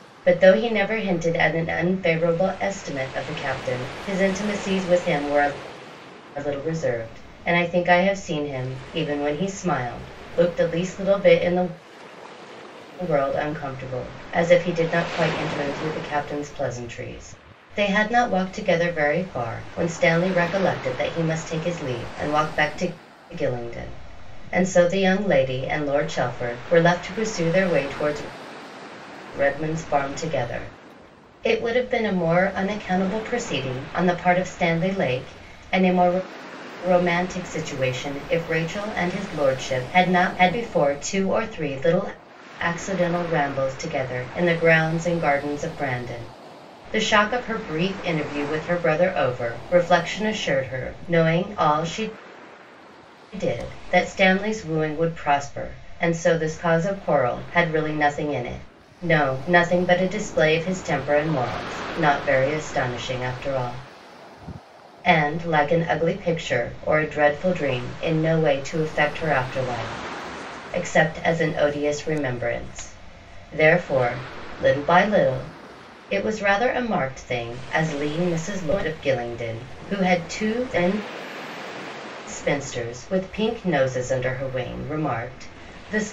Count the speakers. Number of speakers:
one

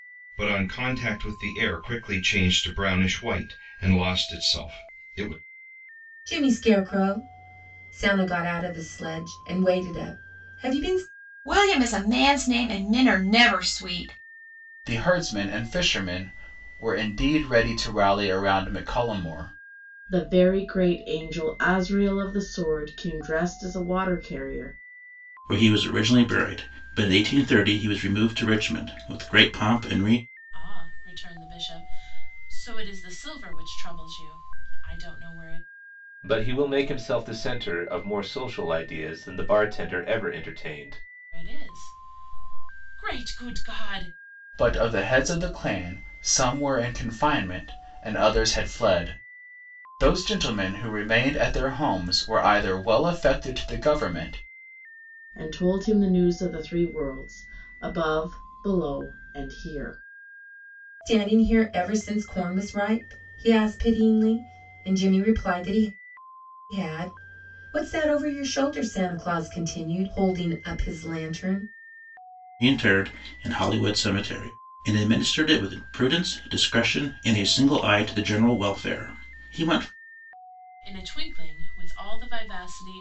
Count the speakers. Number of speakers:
eight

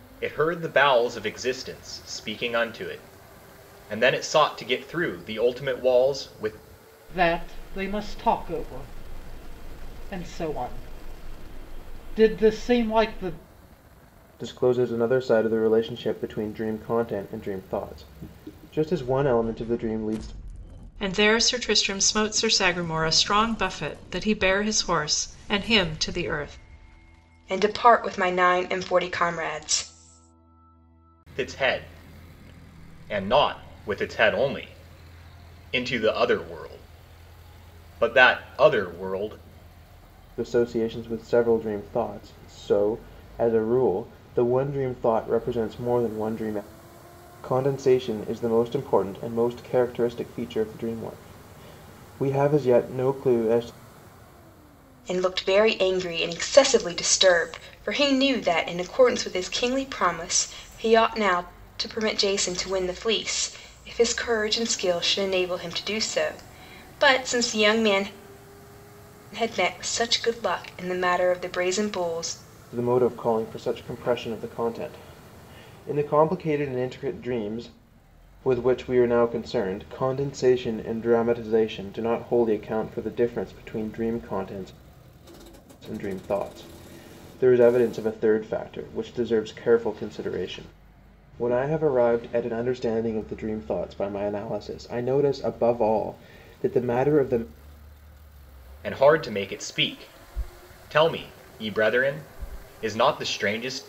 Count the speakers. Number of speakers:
five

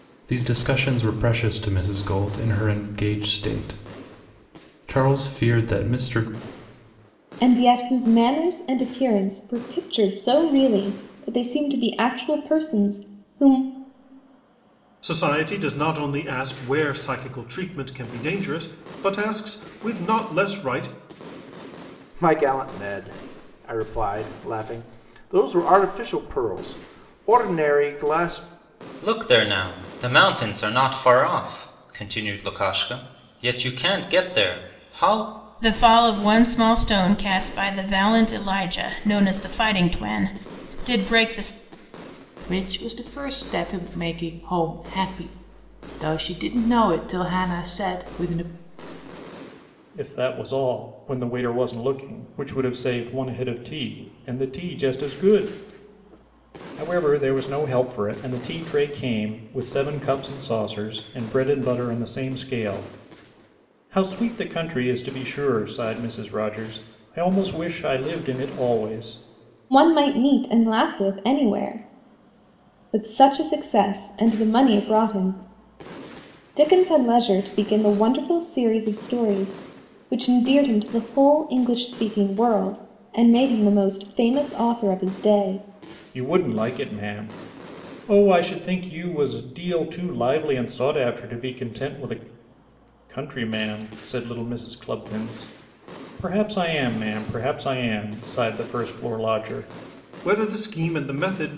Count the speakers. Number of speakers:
eight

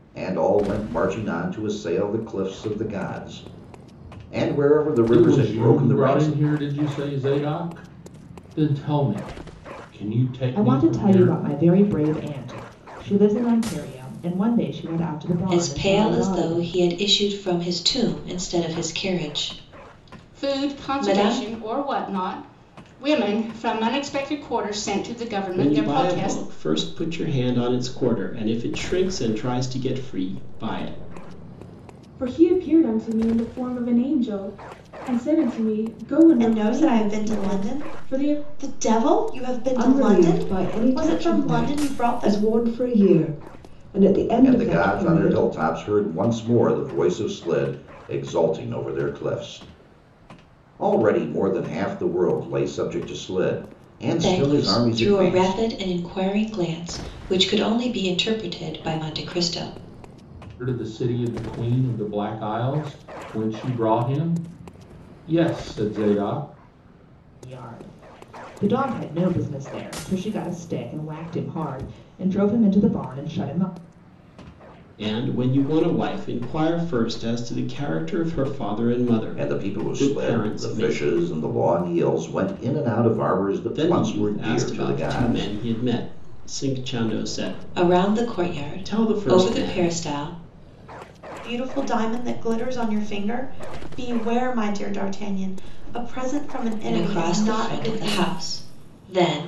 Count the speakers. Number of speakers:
nine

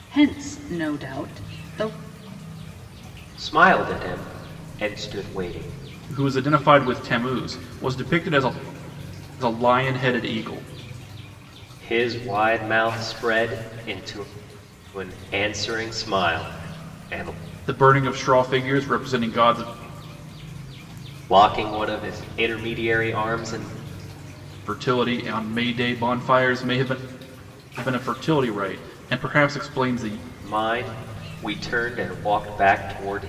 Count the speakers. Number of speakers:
three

